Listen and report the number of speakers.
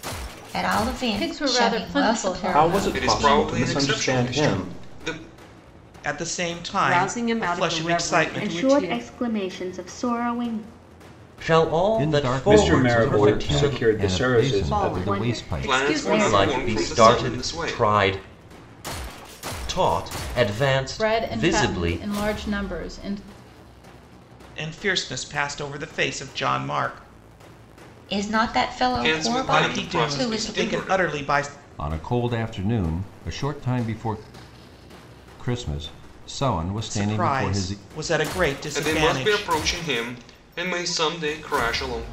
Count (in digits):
10